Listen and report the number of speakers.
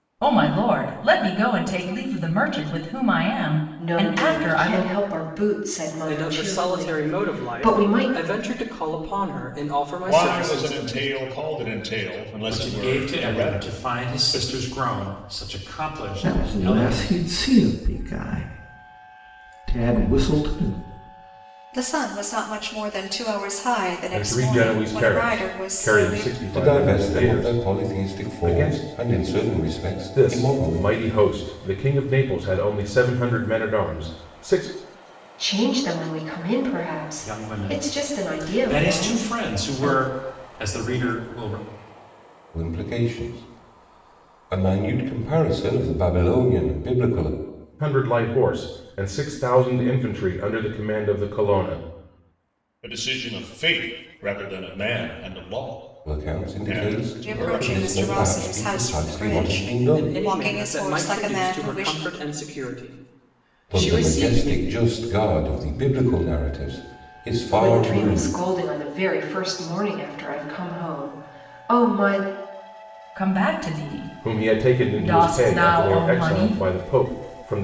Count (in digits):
9